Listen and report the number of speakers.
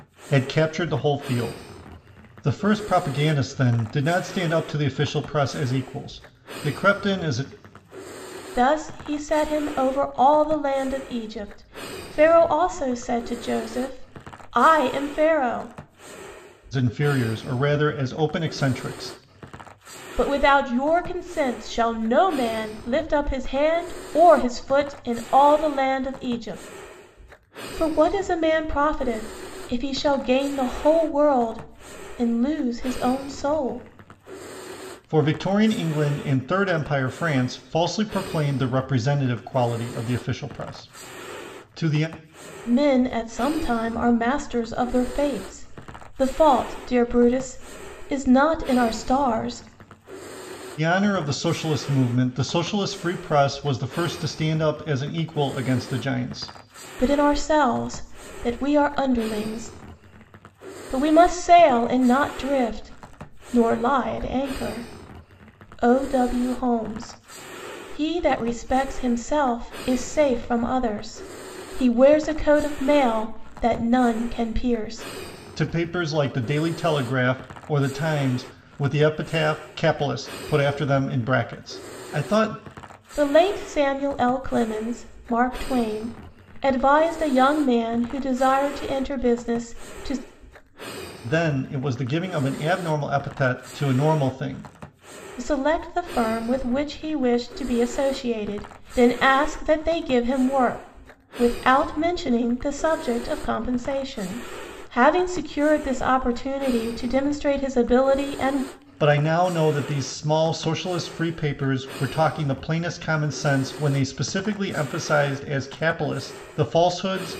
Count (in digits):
2